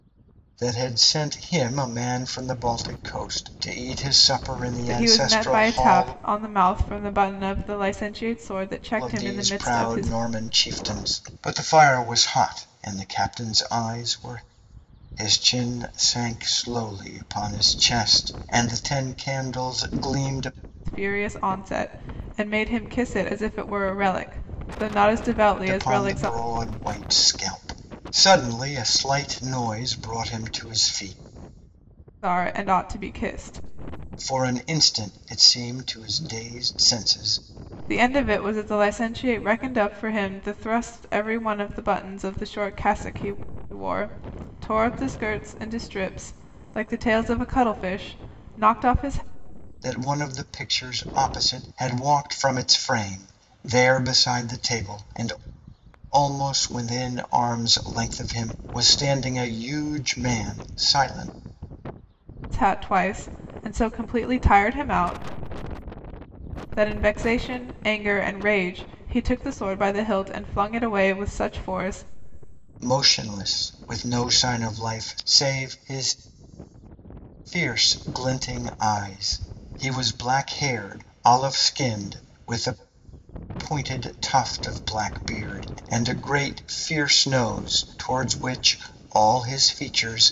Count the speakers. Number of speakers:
2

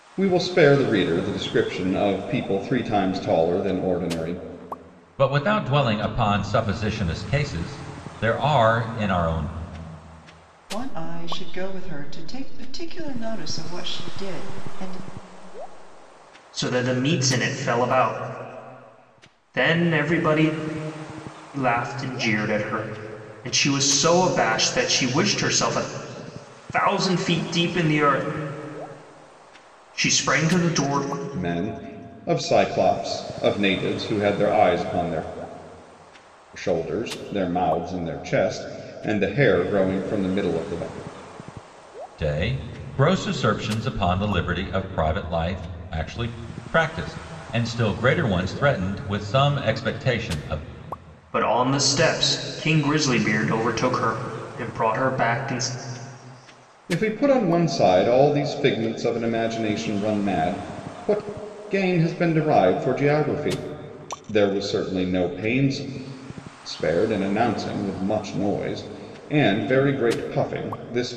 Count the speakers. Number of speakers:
4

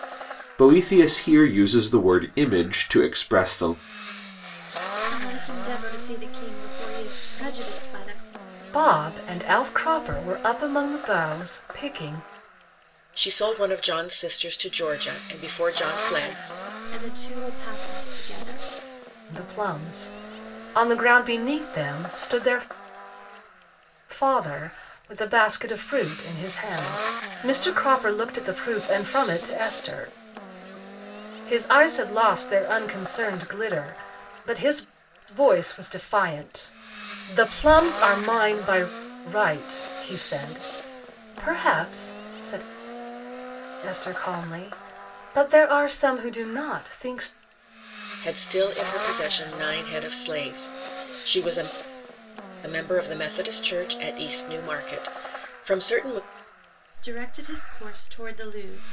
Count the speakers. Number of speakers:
4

